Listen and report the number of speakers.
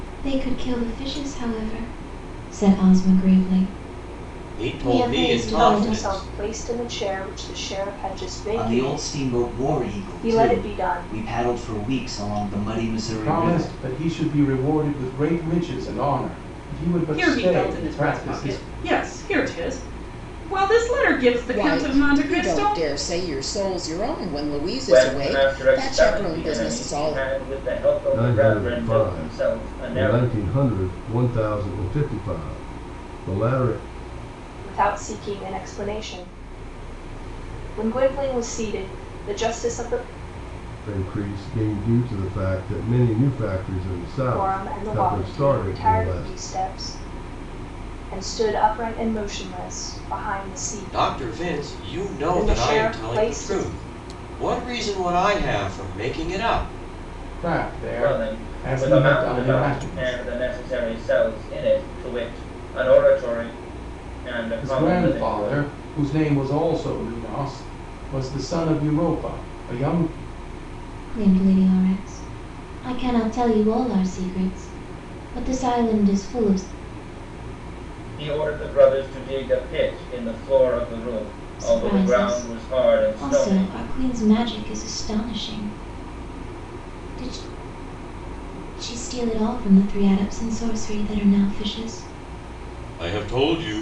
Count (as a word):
nine